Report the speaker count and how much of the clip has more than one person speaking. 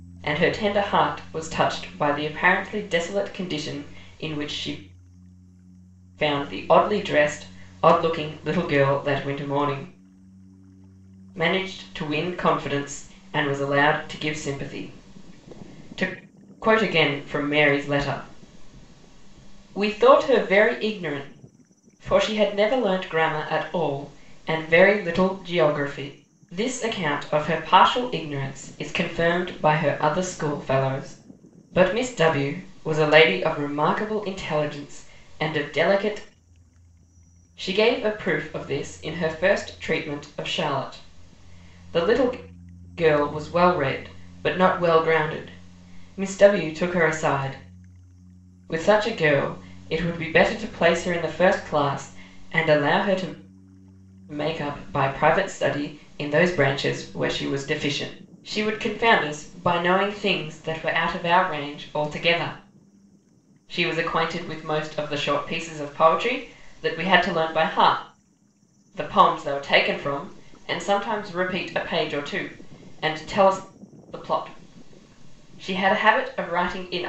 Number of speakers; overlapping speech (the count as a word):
one, no overlap